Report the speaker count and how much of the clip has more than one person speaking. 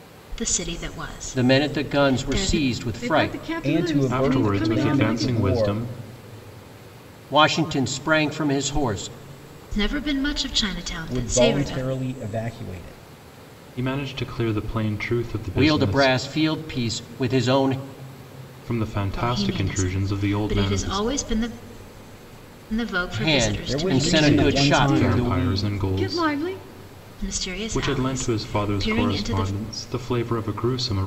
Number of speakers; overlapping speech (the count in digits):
5, about 40%